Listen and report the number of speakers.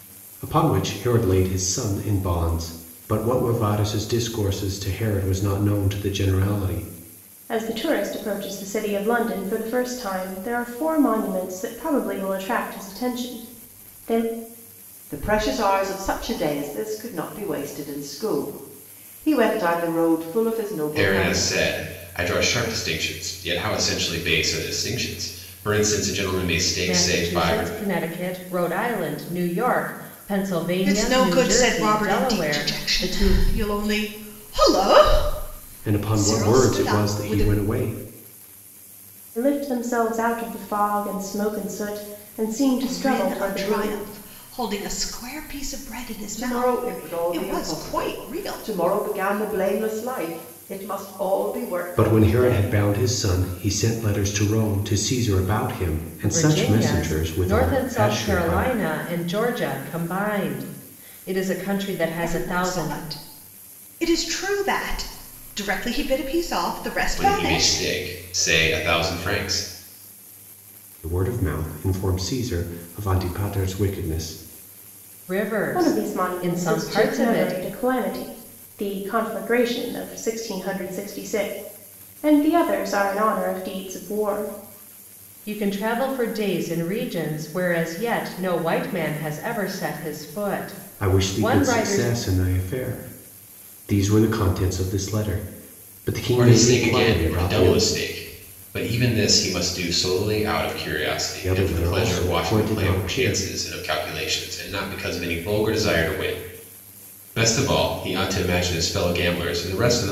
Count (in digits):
6